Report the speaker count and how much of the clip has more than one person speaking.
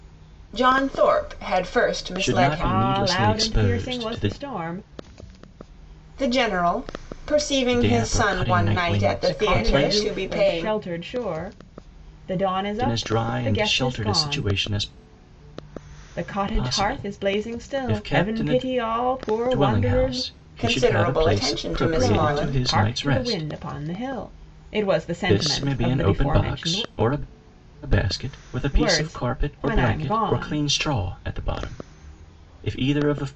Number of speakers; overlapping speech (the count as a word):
three, about 50%